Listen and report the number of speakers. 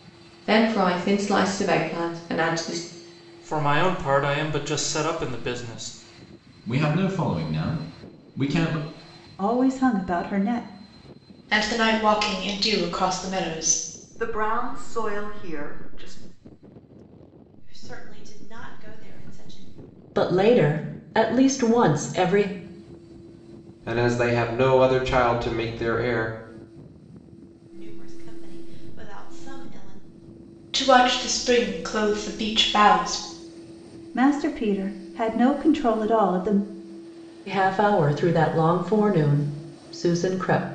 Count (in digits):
9